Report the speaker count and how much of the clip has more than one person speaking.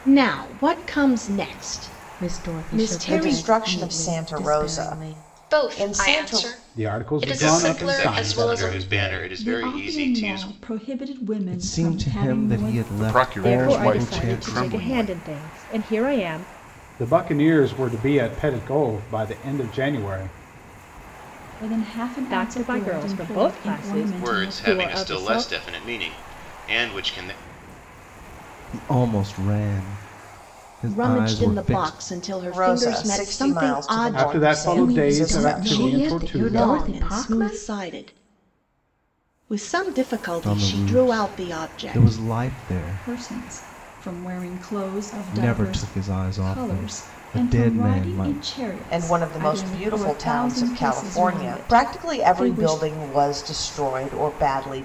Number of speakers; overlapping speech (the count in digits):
10, about 55%